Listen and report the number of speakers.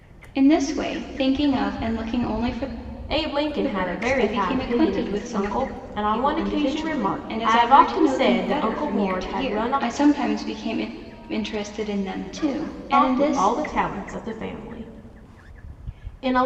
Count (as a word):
two